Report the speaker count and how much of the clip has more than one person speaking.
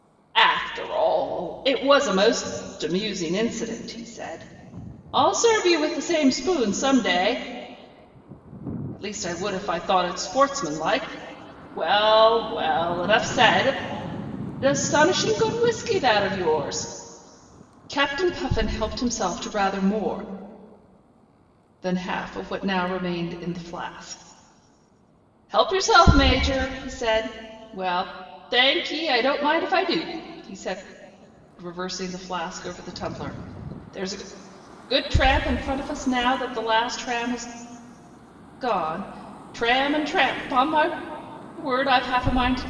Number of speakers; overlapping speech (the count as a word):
one, no overlap